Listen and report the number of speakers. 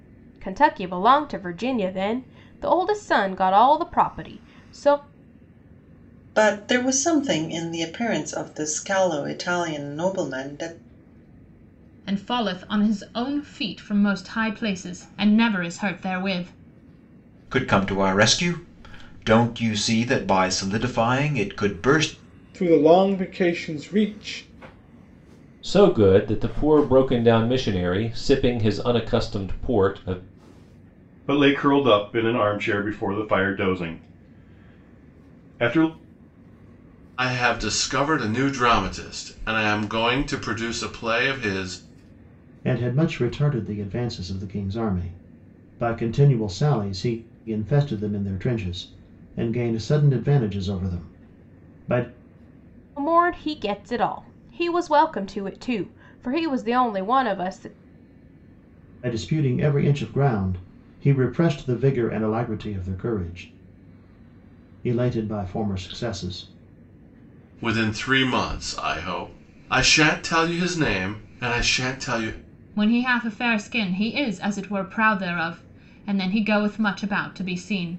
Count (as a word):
nine